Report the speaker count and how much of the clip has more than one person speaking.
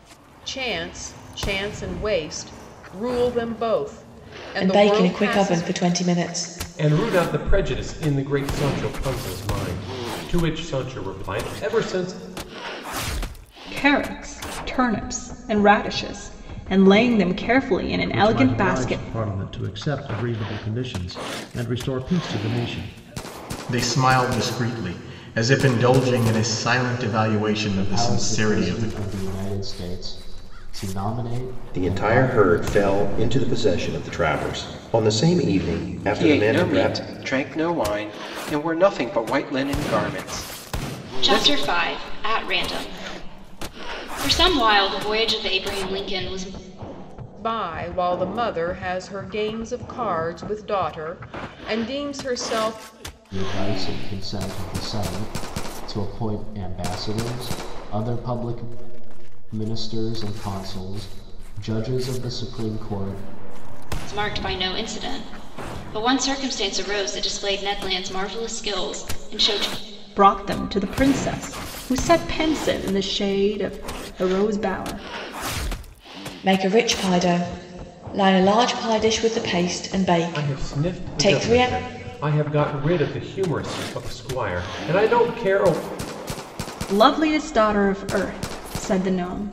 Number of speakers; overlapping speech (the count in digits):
10, about 8%